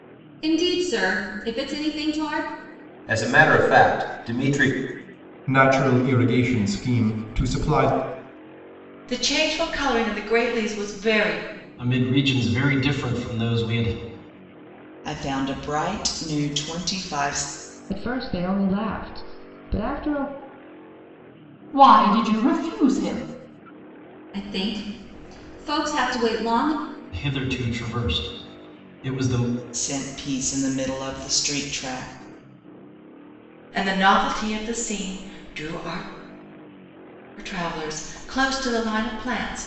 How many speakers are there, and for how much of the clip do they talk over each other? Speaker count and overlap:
8, no overlap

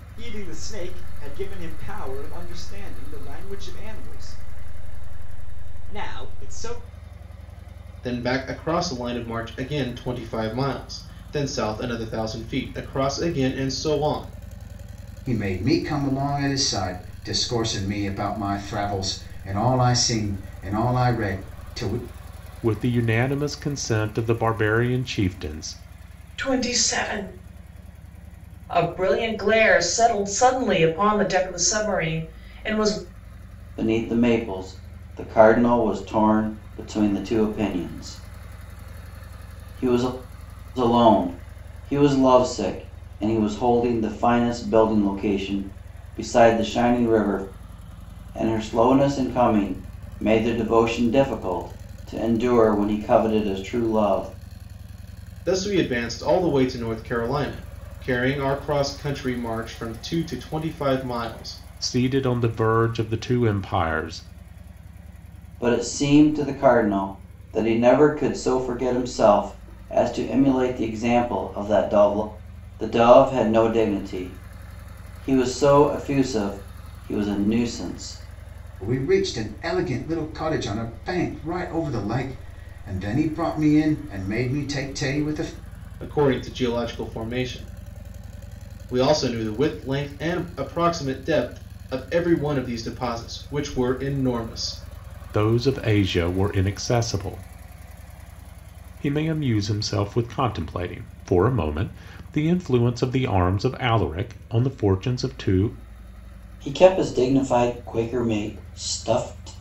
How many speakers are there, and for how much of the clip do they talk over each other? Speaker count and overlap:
6, no overlap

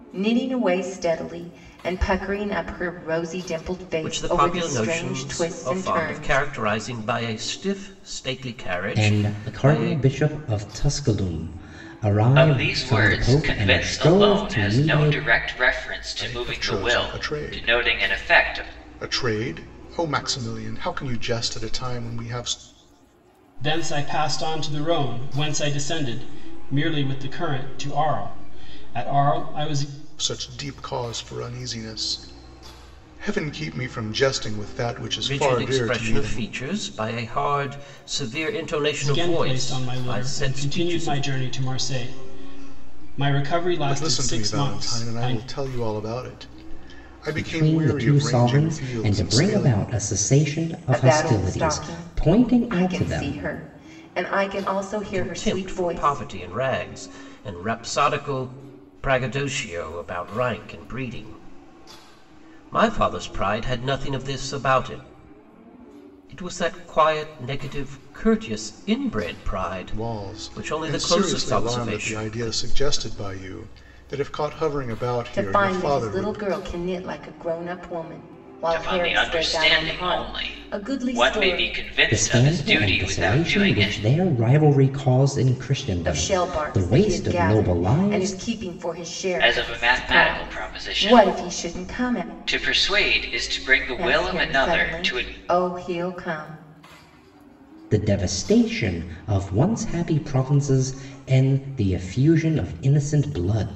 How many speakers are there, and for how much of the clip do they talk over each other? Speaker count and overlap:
6, about 34%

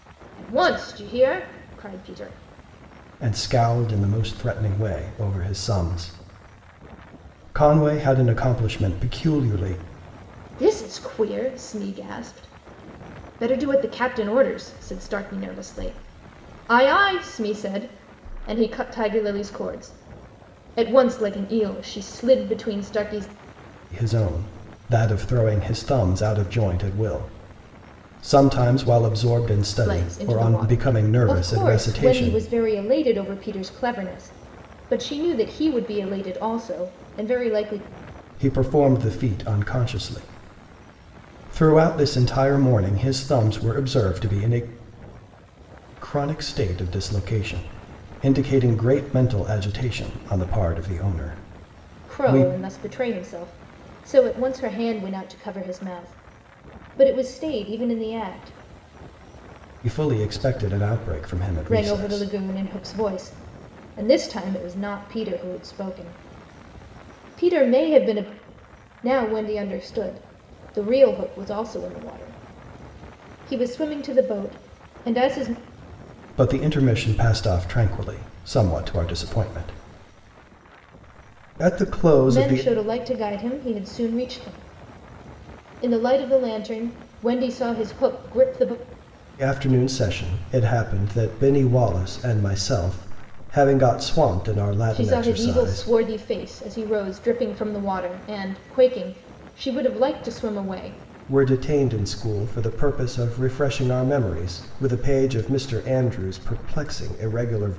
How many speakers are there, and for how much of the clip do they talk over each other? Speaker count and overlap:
2, about 4%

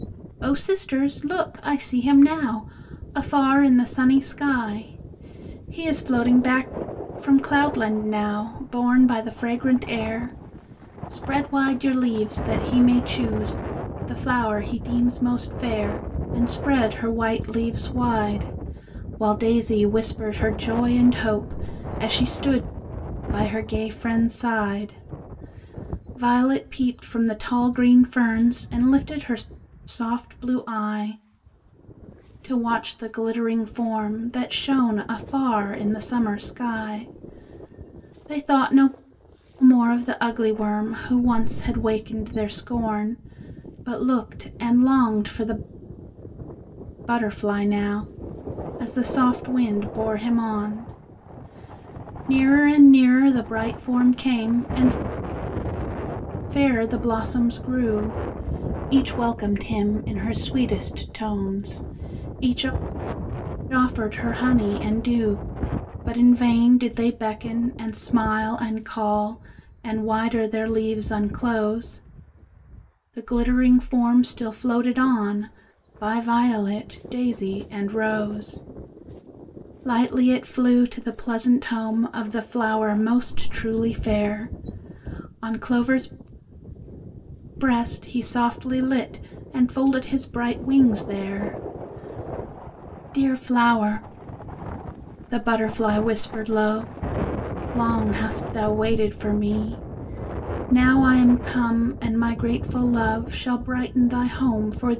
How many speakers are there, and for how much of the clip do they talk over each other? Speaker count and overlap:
1, no overlap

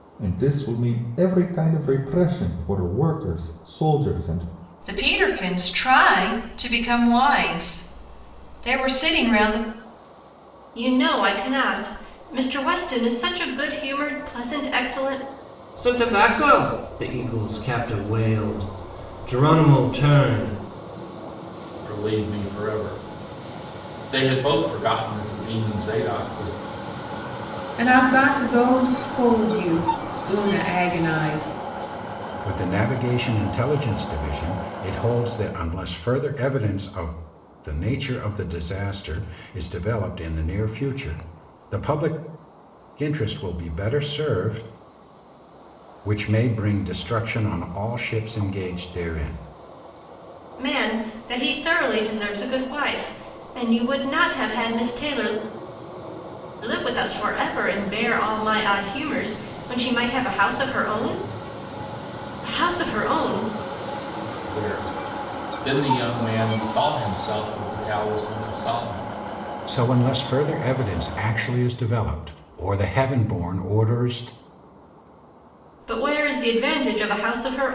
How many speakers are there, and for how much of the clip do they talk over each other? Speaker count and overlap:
7, no overlap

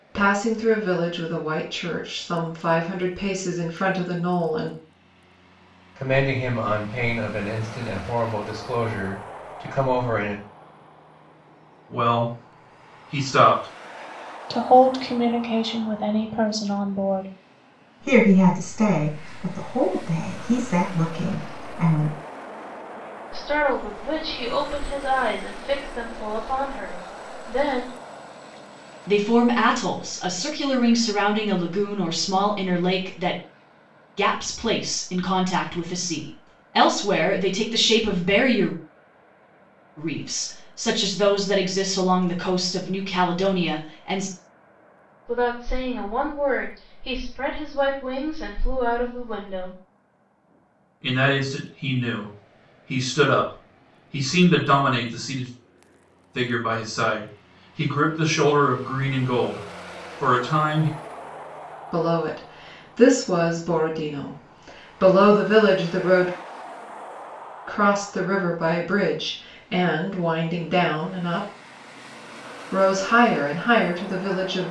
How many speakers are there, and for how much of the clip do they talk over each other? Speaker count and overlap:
7, no overlap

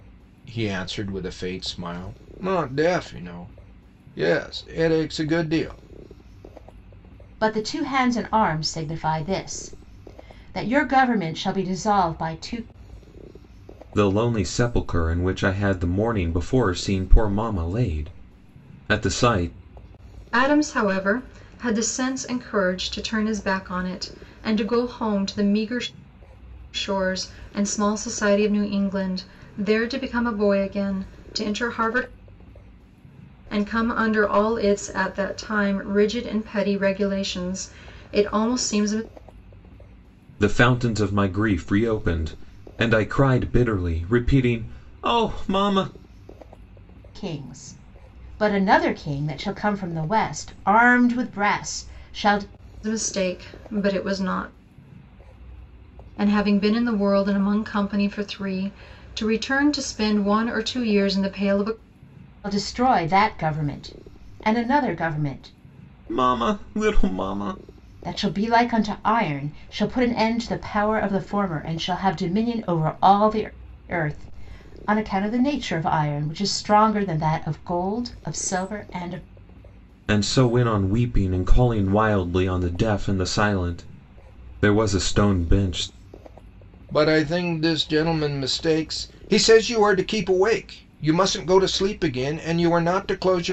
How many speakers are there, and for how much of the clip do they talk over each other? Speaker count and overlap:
4, no overlap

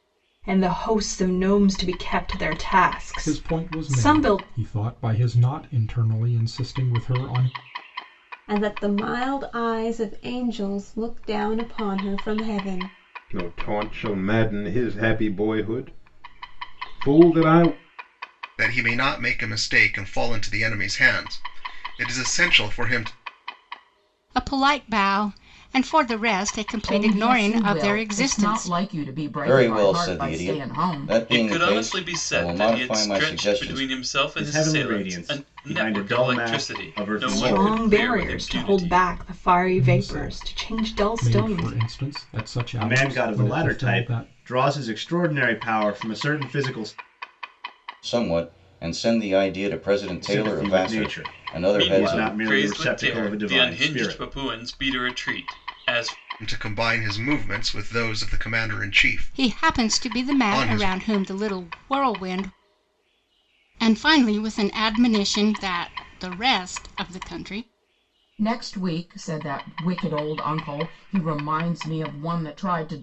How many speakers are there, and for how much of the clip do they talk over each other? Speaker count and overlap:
10, about 29%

